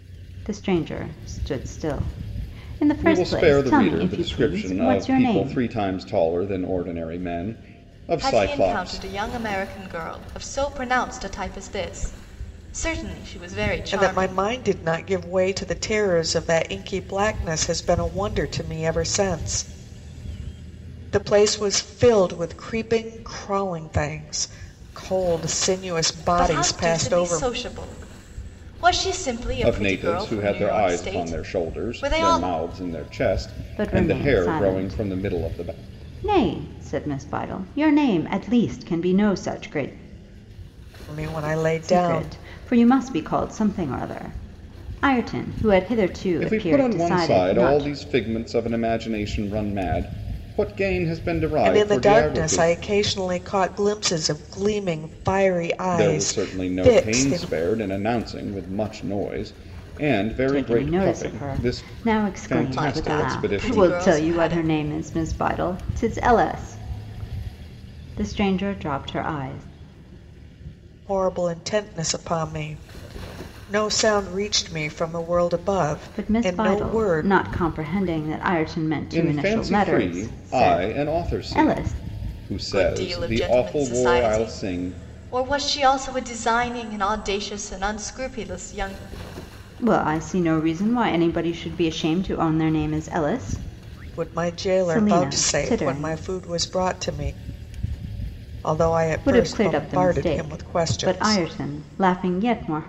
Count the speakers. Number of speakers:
four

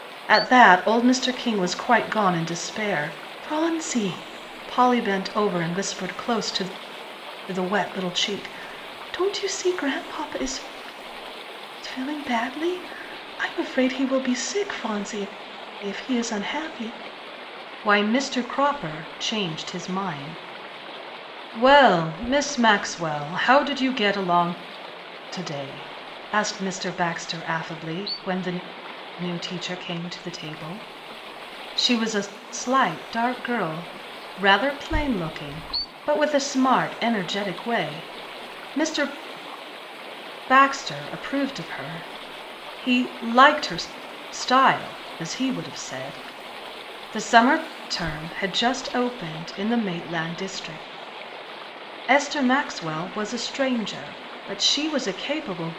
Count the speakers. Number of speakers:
one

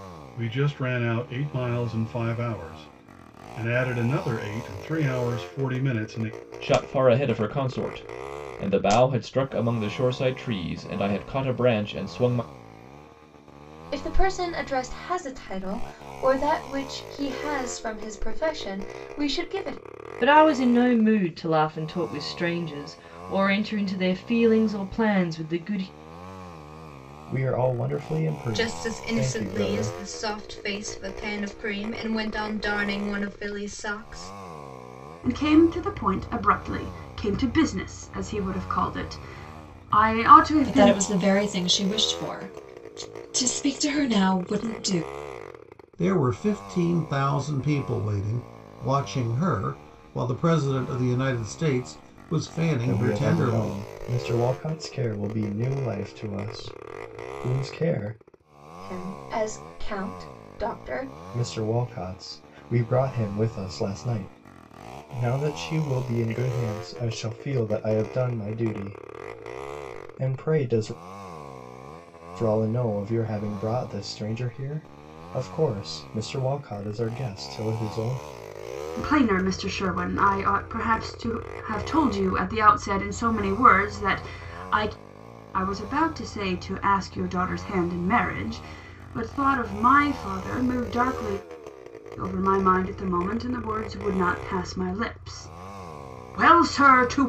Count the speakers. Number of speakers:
nine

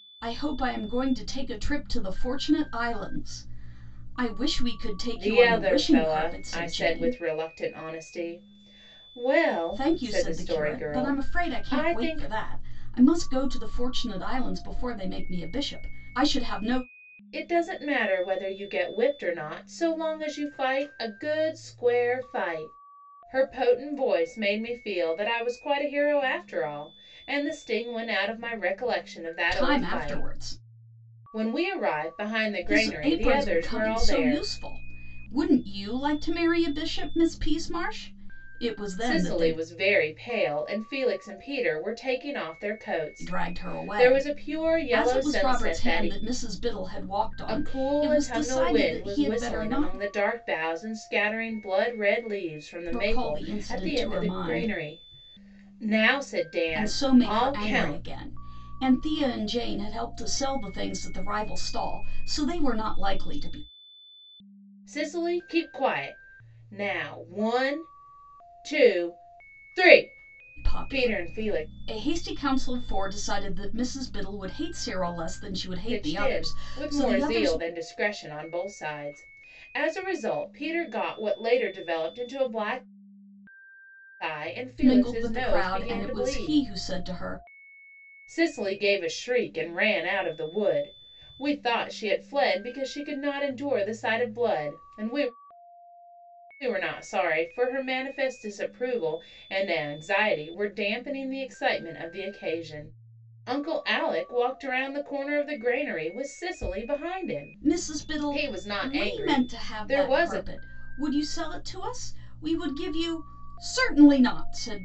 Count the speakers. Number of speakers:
two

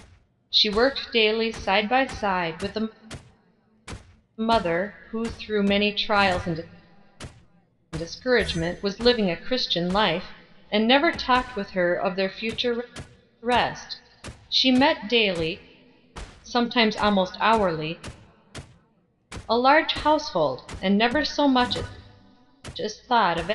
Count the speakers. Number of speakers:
one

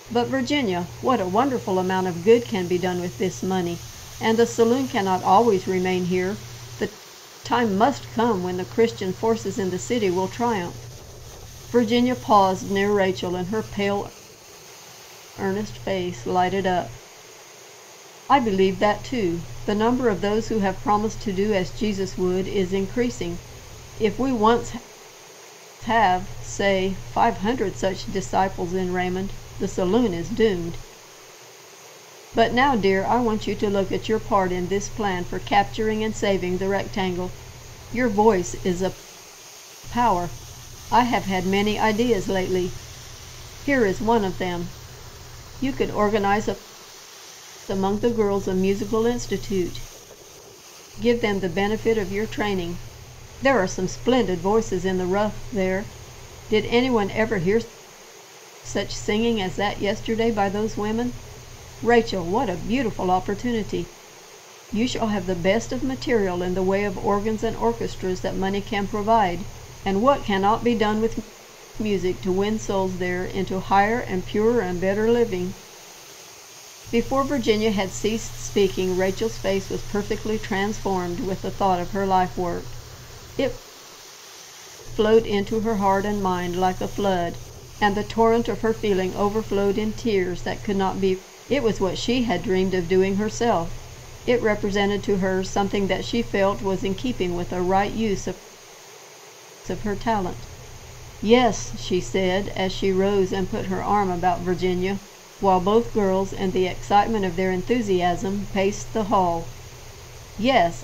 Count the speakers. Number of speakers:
one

